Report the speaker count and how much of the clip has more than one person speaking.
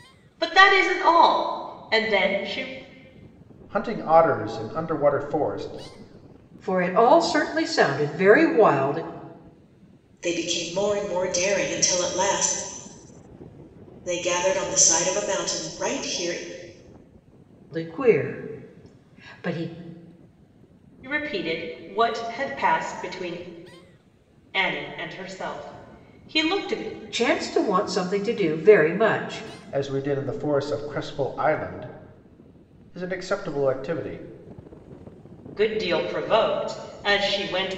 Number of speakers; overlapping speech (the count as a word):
four, no overlap